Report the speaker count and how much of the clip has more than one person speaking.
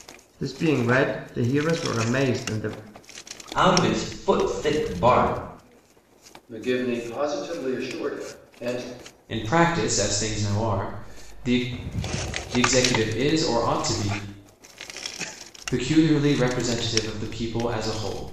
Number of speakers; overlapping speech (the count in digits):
4, no overlap